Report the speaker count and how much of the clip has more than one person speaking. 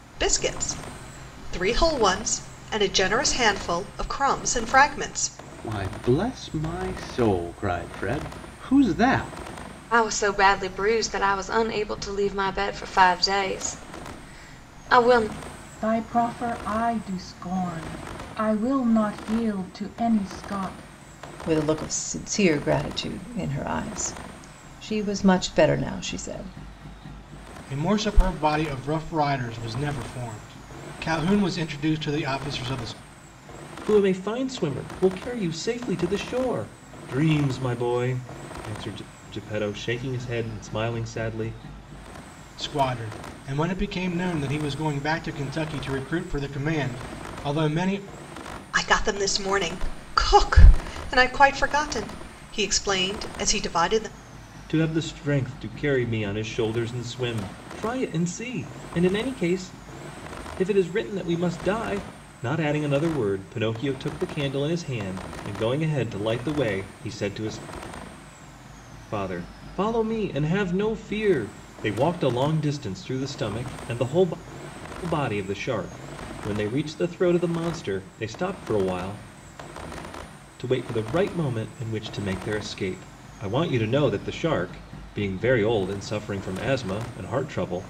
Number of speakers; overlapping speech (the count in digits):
7, no overlap